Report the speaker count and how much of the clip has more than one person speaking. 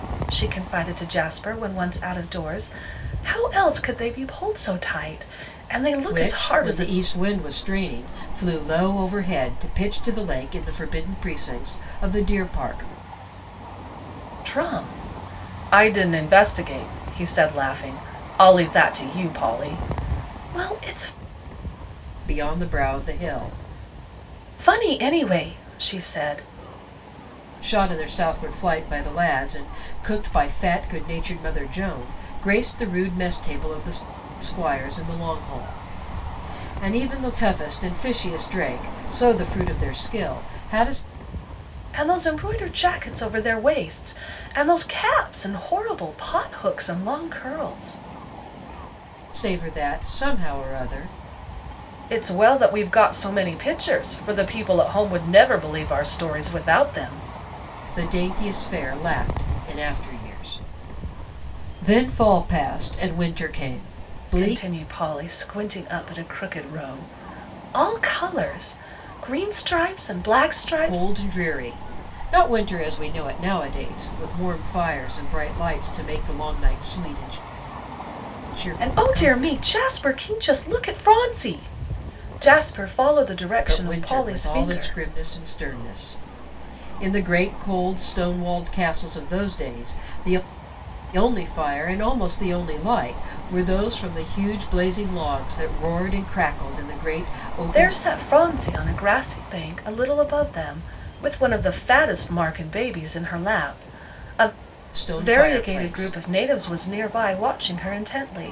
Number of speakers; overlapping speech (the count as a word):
two, about 5%